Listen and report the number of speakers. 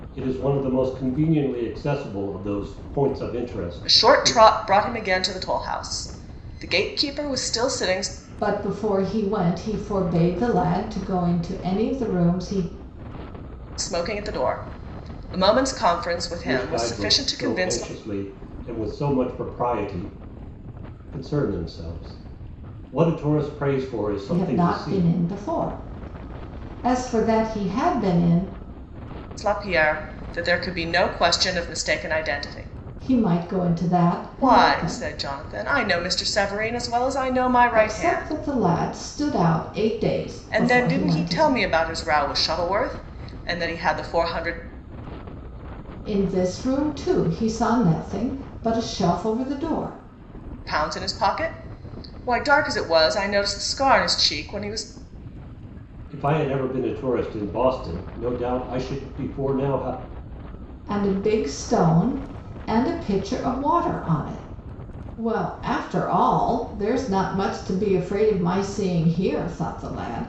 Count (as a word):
three